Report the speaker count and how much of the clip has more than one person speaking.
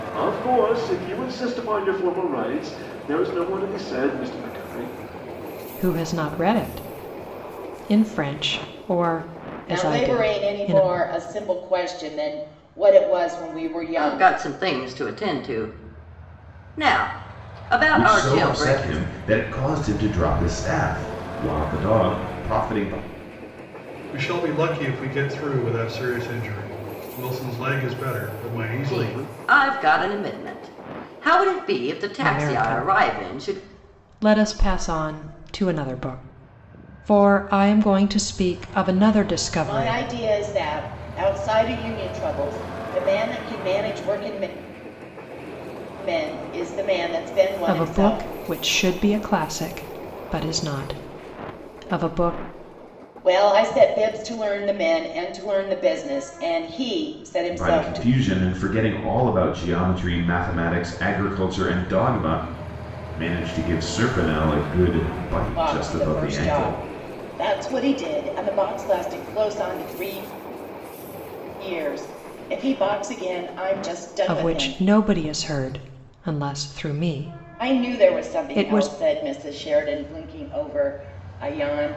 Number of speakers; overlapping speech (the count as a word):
six, about 12%